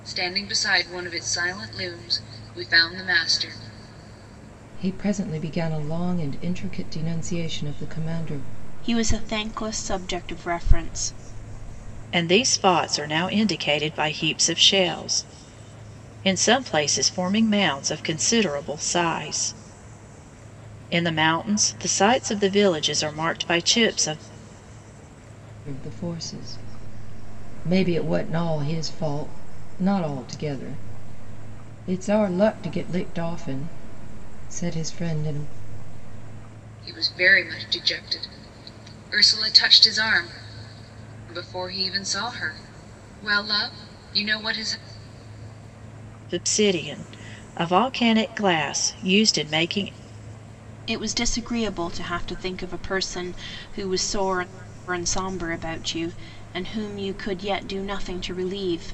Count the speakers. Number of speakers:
4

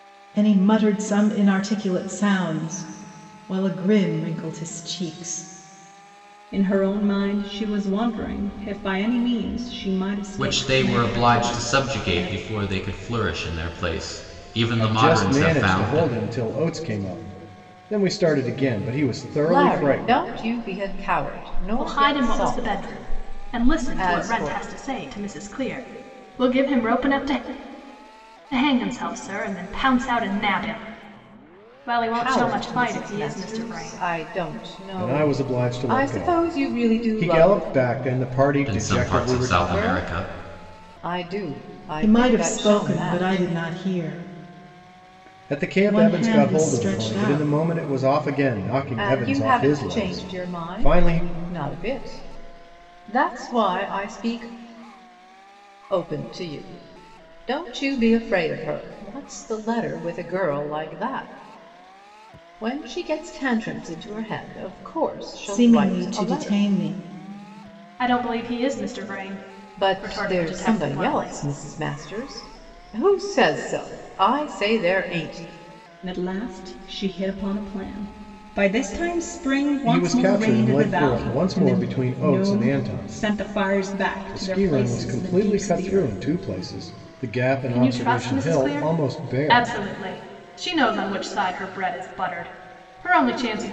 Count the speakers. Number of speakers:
6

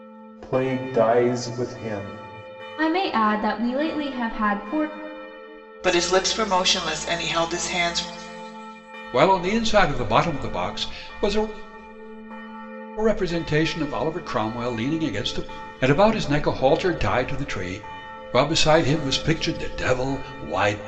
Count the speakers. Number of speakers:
4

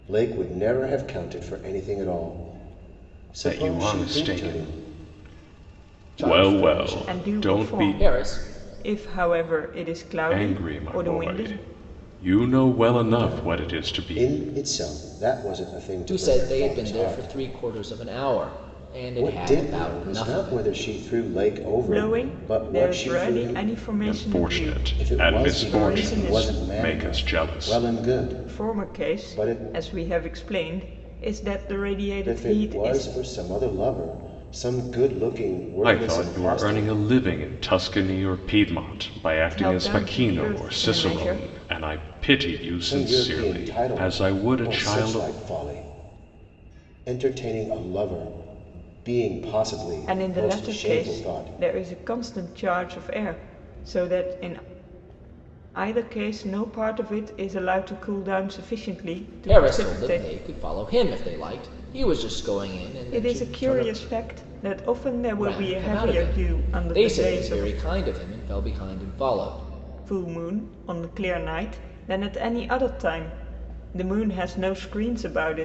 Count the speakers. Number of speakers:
4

